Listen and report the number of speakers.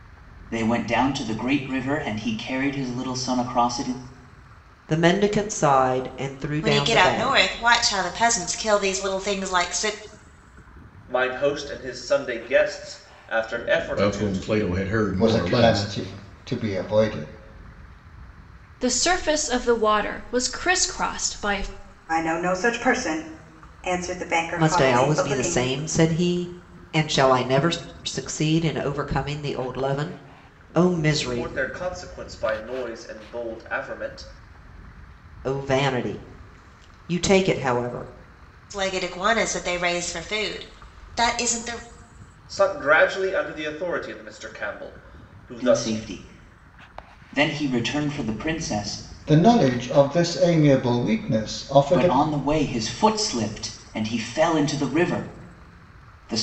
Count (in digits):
8